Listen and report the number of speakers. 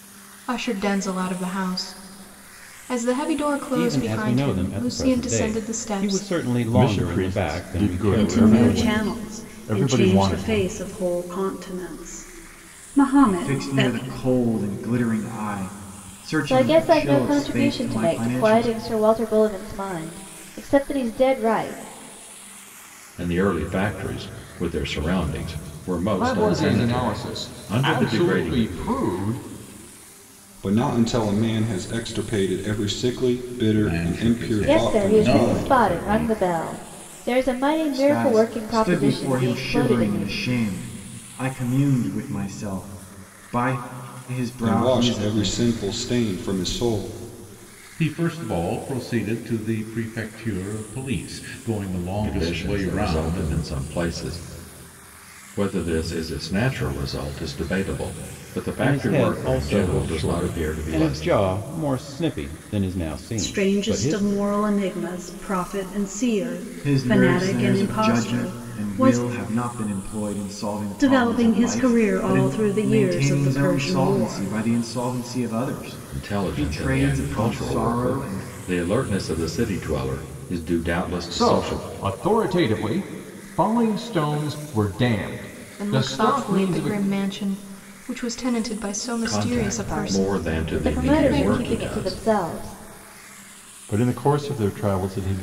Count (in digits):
10